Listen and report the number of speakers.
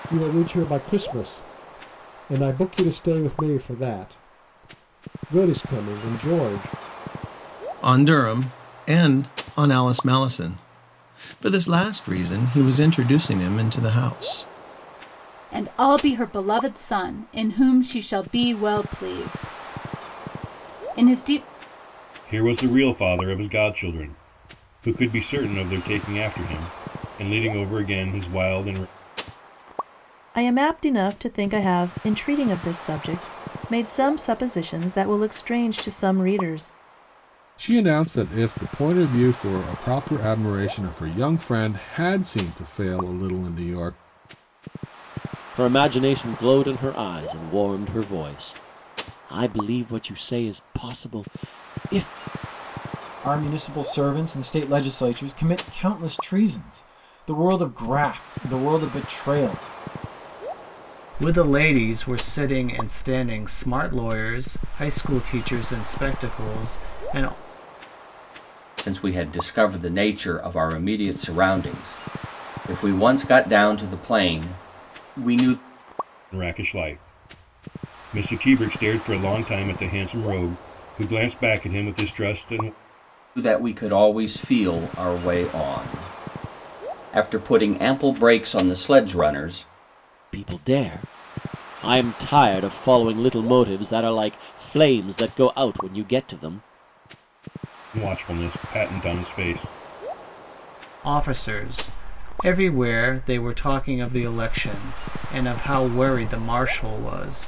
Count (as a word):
ten